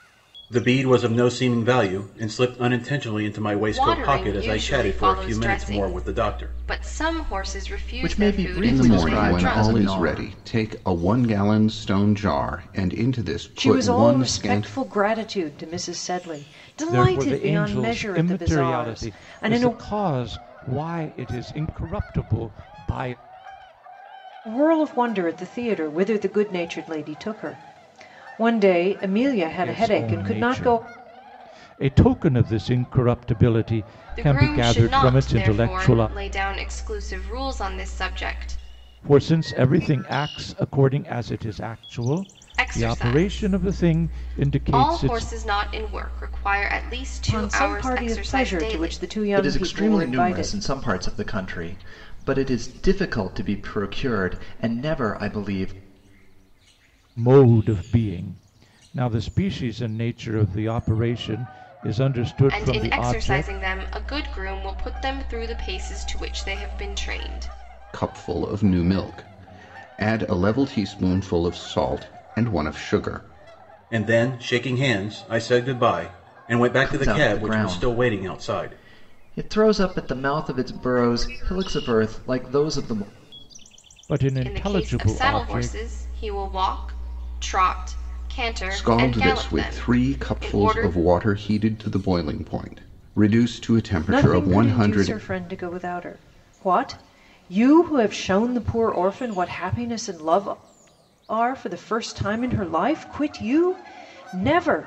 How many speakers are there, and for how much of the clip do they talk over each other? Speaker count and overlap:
6, about 25%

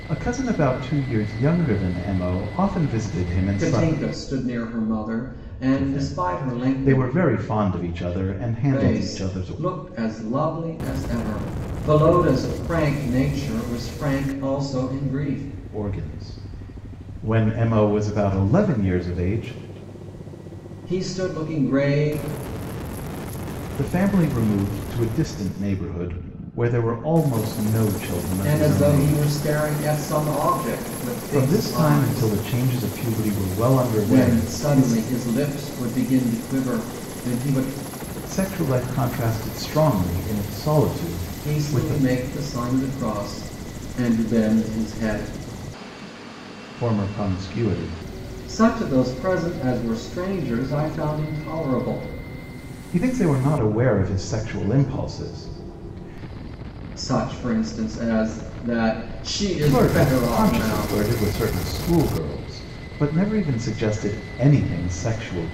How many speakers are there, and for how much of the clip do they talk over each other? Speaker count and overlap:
2, about 12%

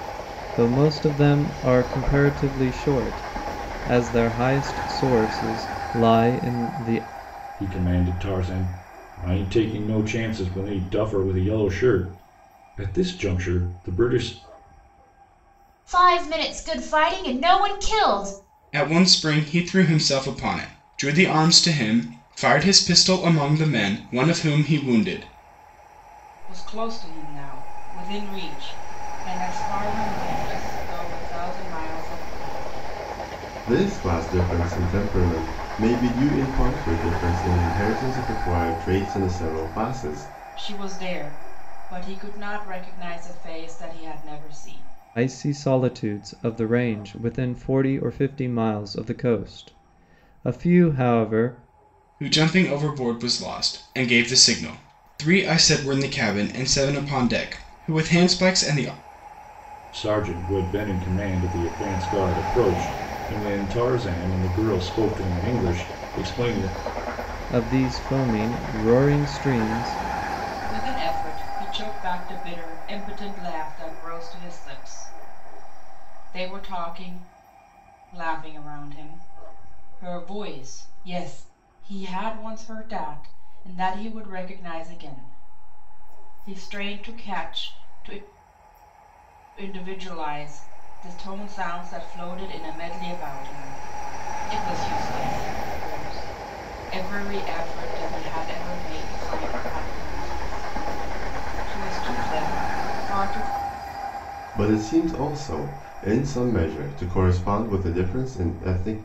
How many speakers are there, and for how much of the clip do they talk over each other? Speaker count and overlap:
6, no overlap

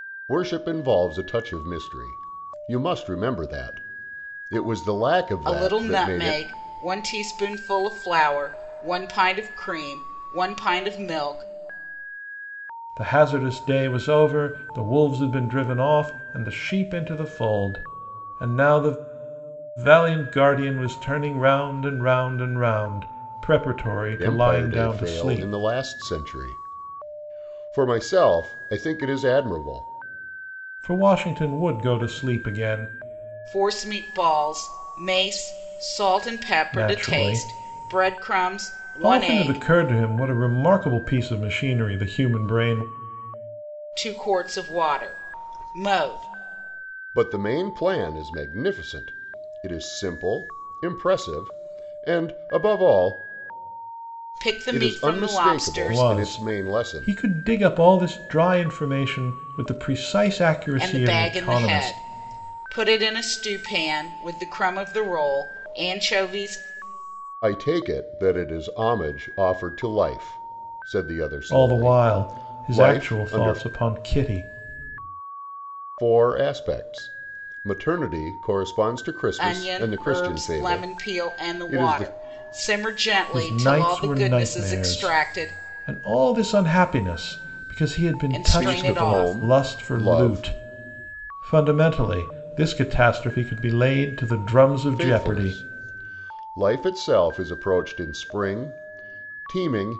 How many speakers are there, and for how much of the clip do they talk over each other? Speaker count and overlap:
3, about 19%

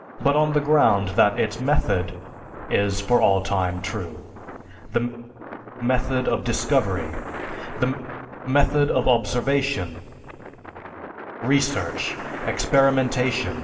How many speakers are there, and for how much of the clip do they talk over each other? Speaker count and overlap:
1, no overlap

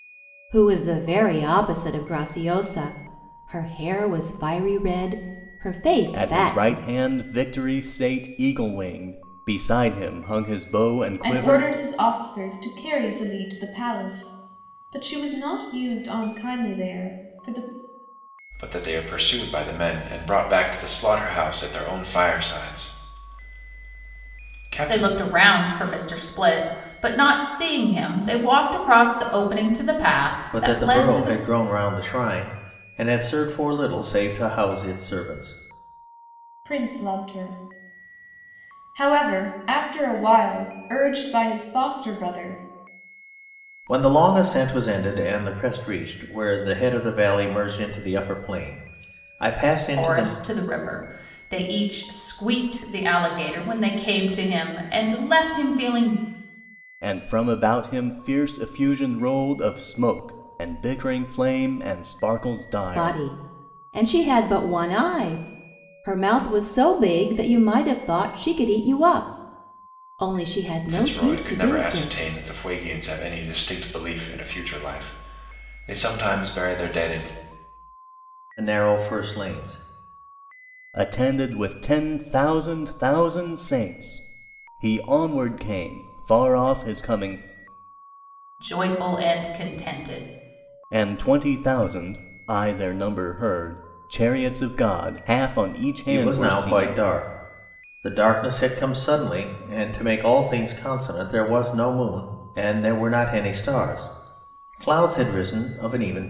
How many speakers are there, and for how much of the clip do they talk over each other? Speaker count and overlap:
6, about 5%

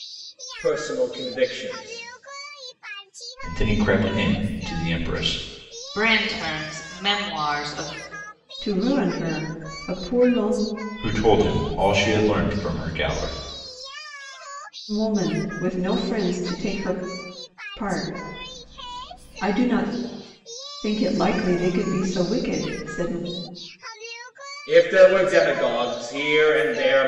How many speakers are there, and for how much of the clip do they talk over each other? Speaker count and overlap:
4, no overlap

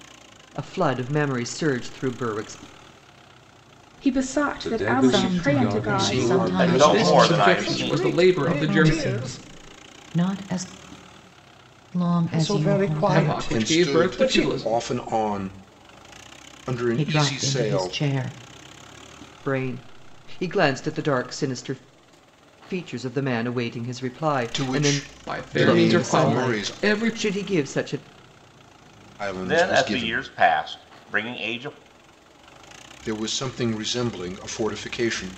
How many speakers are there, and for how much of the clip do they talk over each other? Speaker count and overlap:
8, about 34%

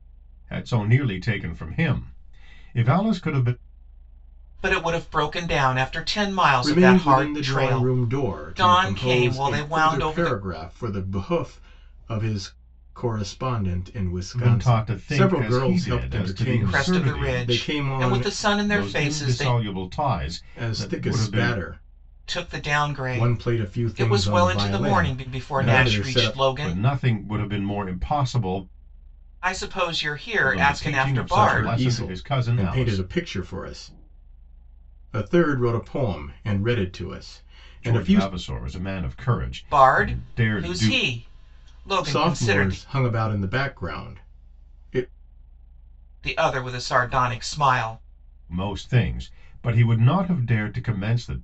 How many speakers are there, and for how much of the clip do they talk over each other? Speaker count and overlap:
3, about 36%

